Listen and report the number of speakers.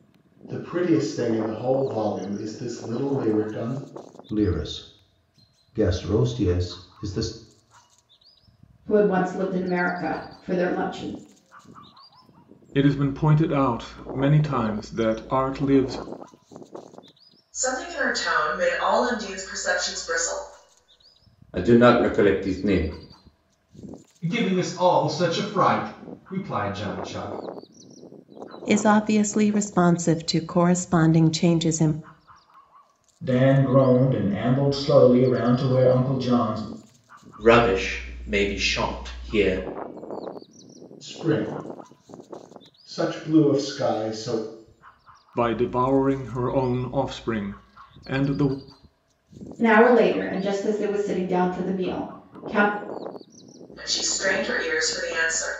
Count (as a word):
ten